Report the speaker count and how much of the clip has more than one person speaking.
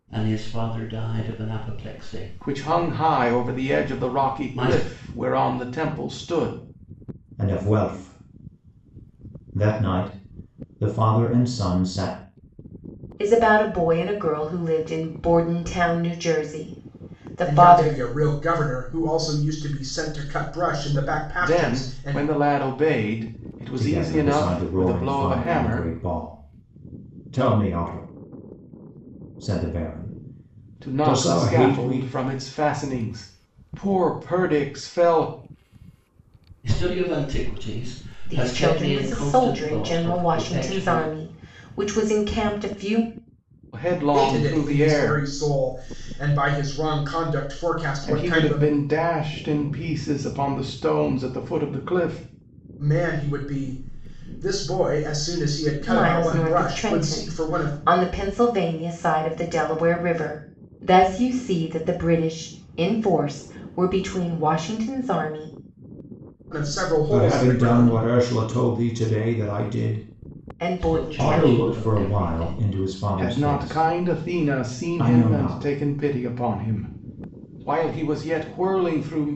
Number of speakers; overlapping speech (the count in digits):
5, about 24%